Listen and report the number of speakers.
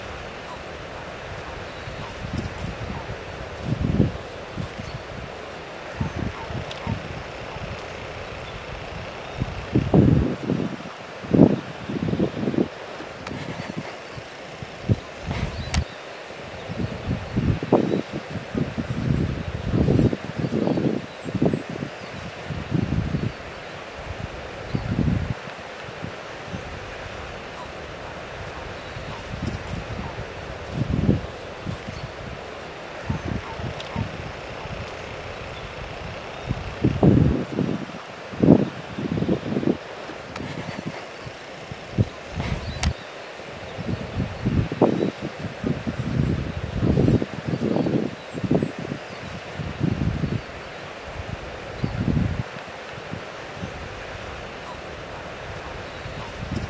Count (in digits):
0